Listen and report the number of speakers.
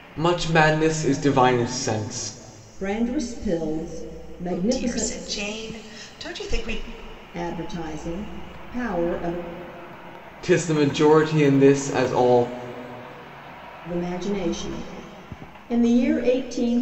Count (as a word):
three